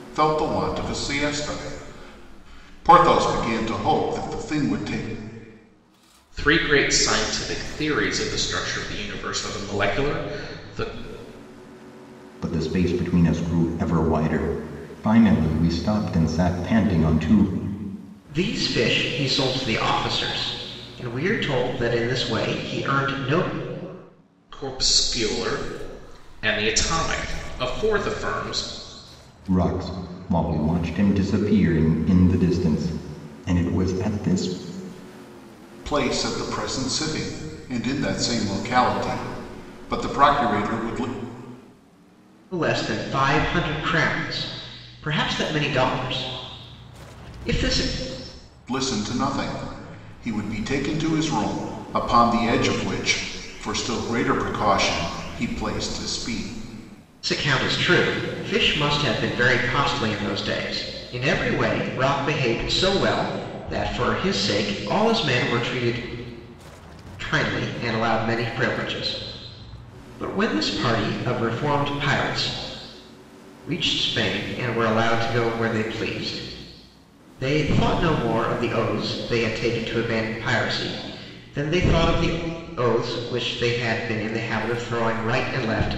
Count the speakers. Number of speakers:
4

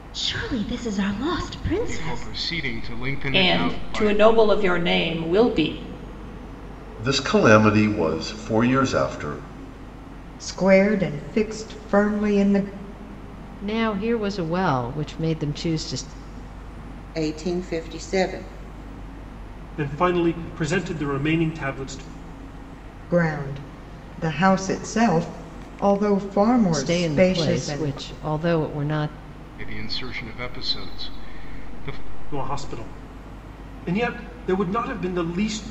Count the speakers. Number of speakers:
8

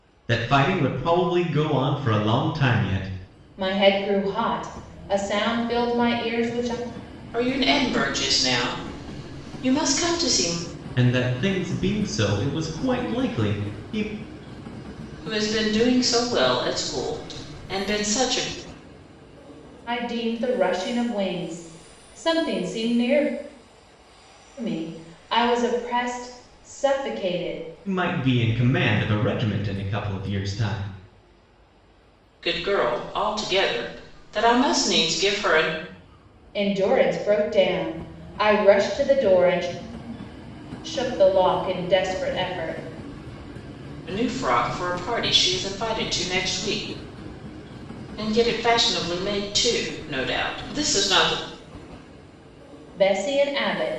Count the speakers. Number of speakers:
3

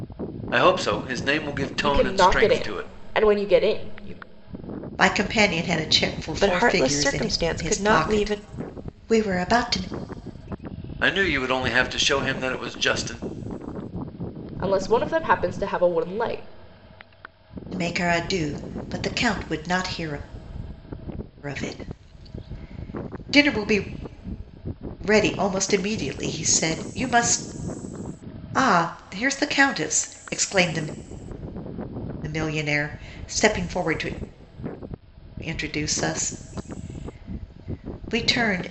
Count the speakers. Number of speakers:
4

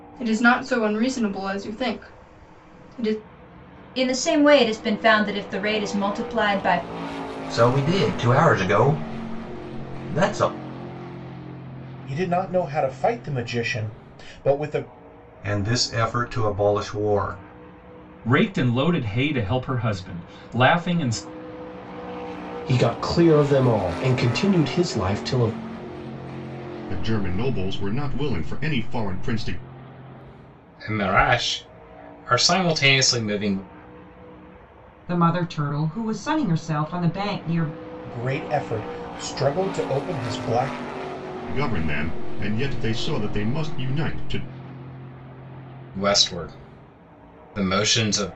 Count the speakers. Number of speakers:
10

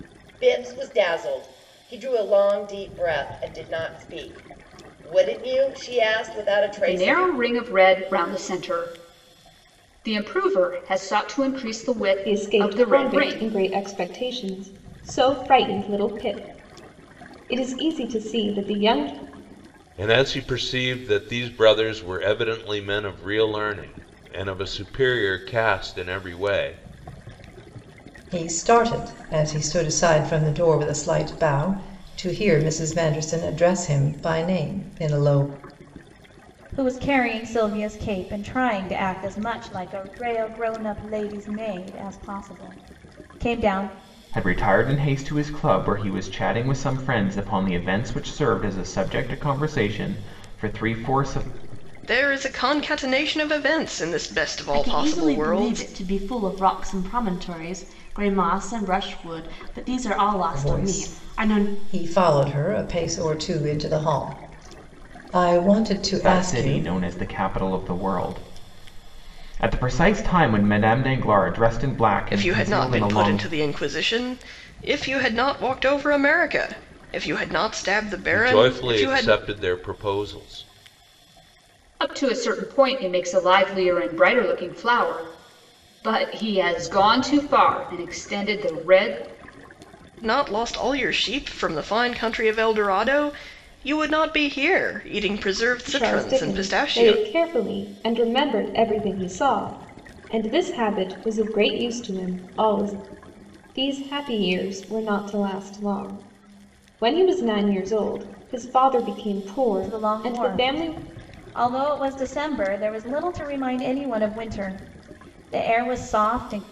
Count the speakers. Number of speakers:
9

